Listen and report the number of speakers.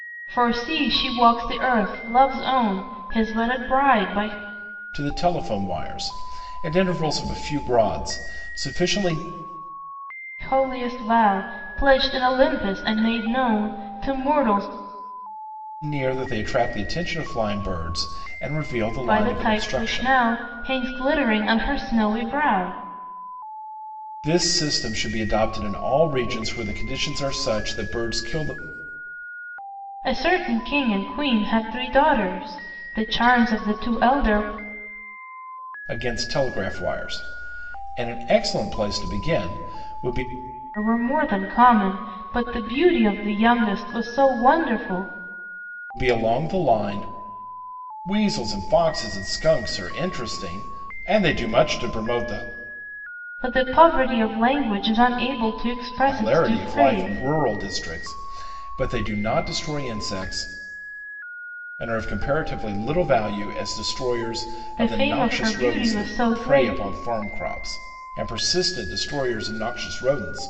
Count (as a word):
two